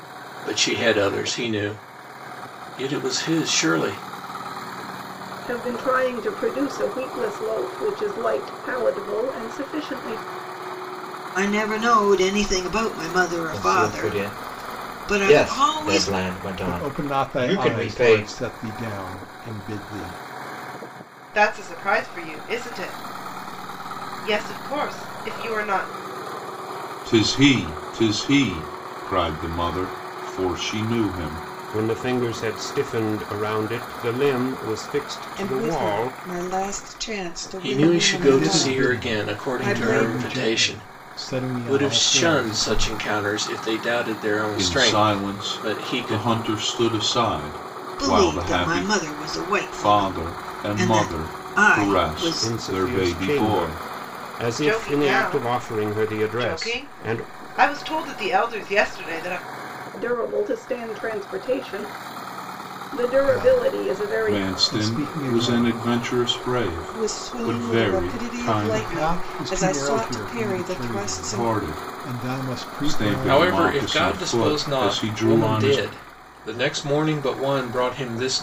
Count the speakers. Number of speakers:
nine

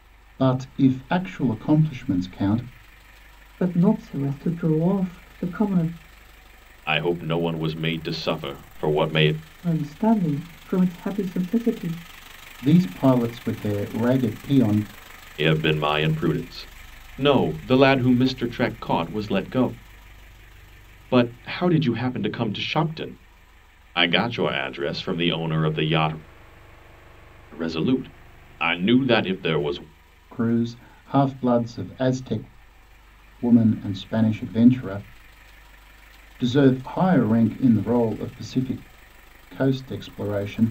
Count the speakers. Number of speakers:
three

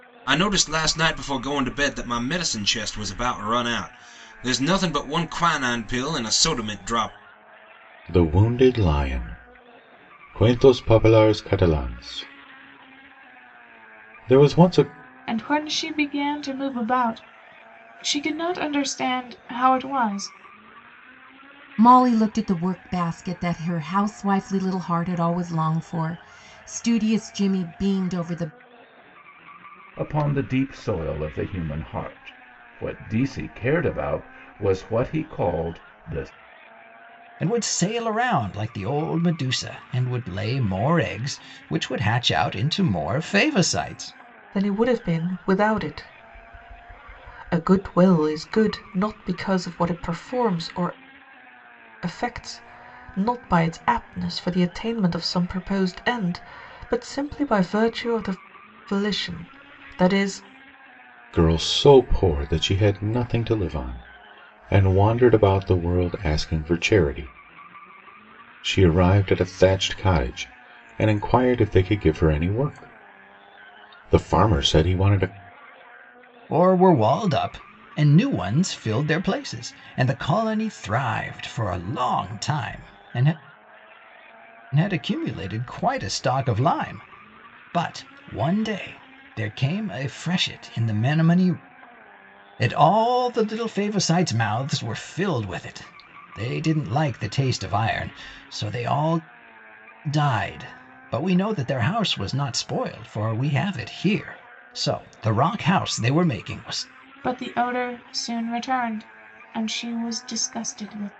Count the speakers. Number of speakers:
seven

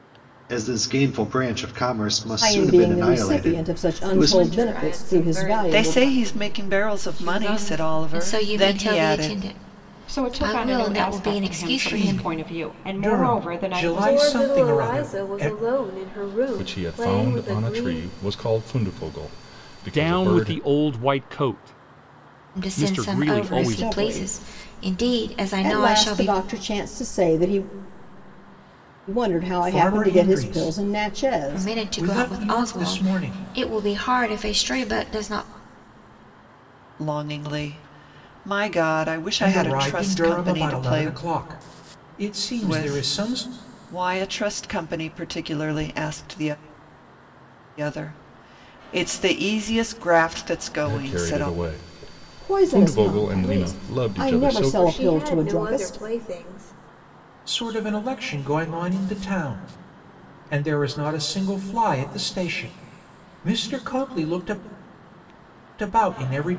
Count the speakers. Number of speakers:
ten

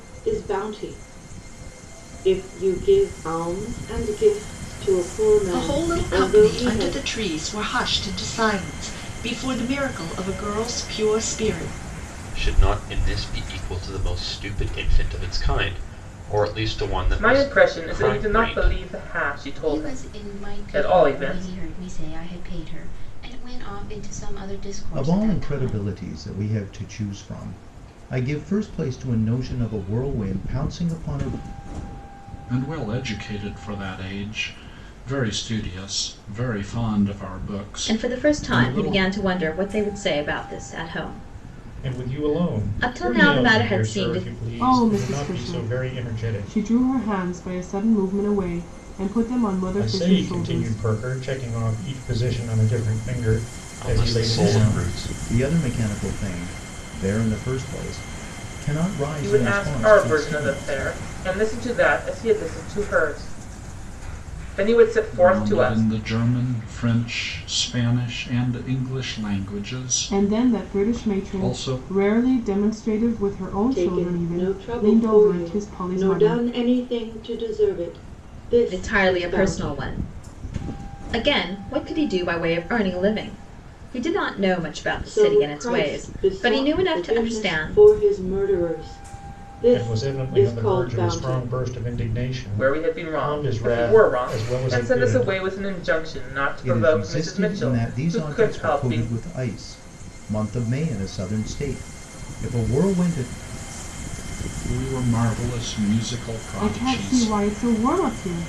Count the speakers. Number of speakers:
ten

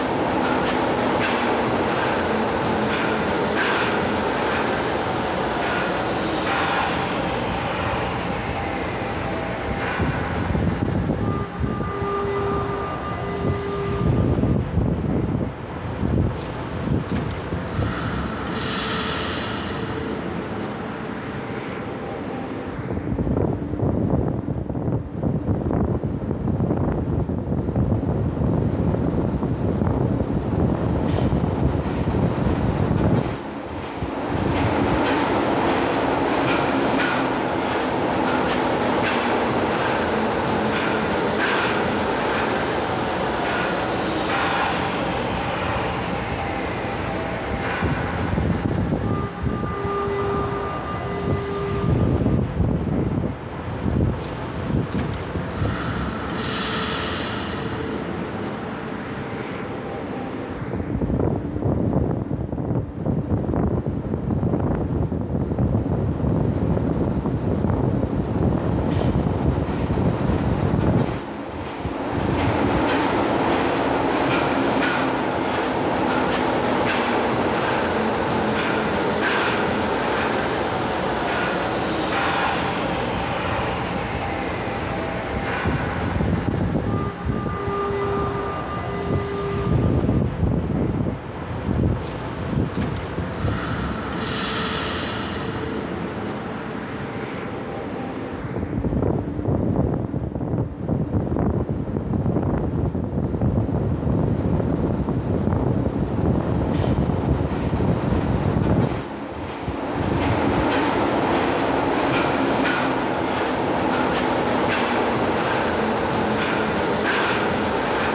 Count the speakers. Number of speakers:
zero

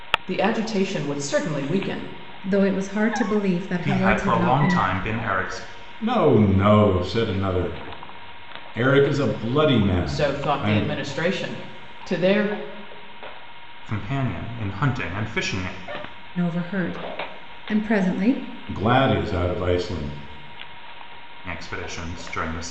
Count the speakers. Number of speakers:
four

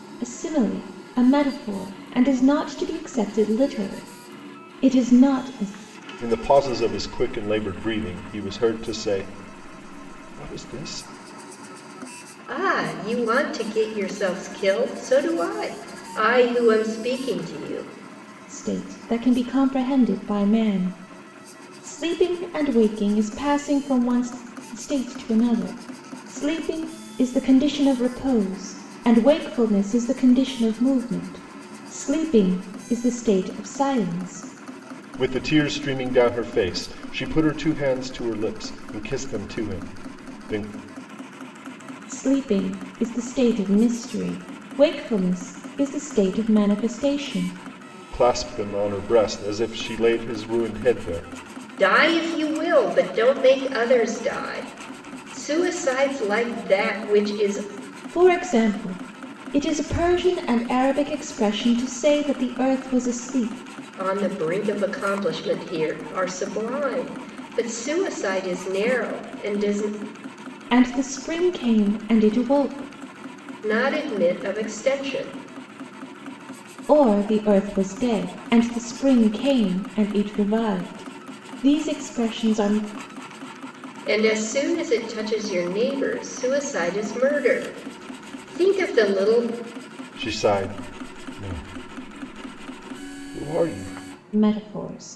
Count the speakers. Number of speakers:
three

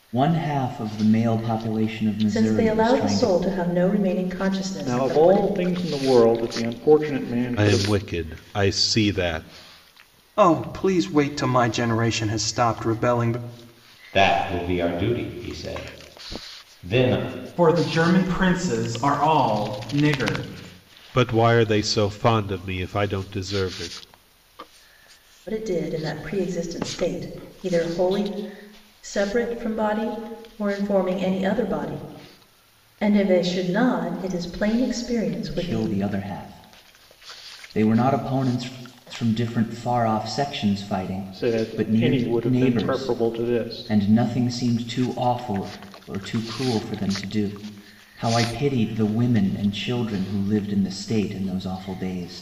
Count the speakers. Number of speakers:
seven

